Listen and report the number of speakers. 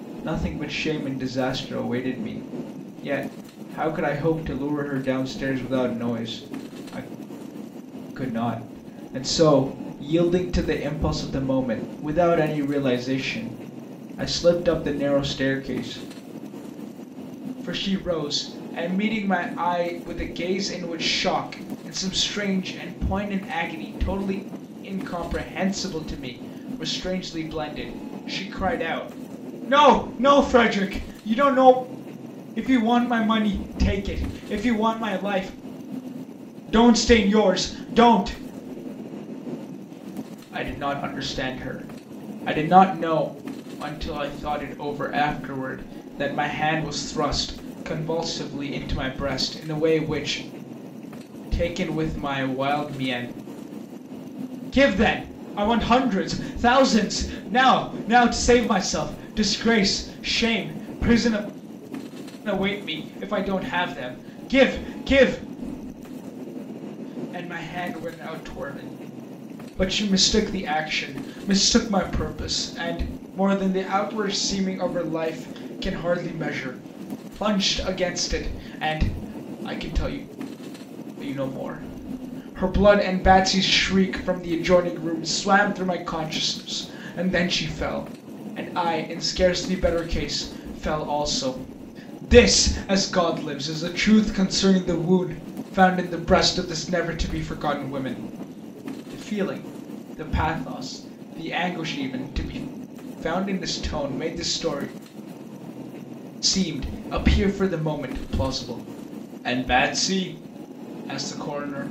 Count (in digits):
1